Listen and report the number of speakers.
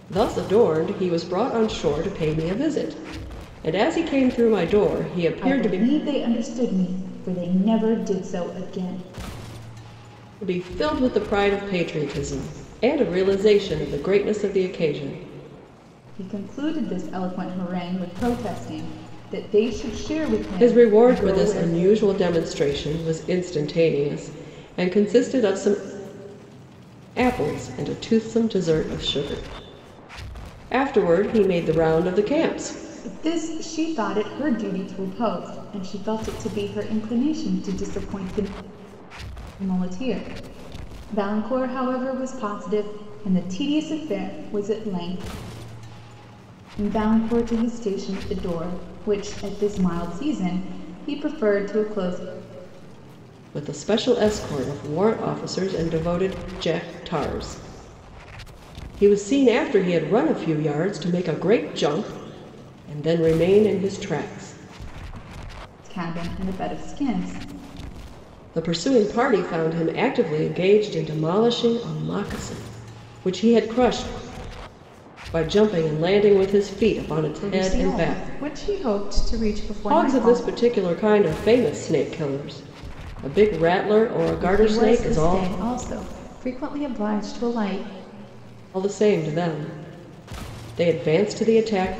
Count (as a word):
two